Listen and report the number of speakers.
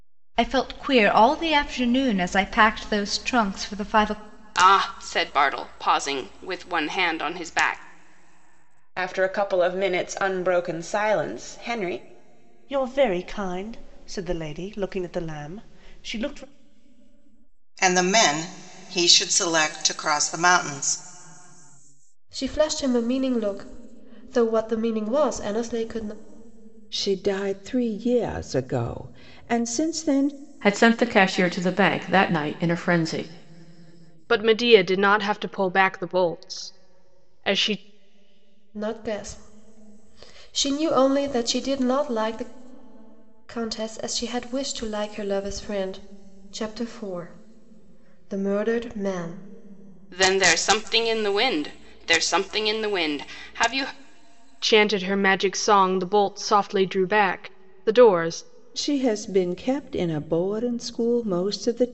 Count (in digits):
9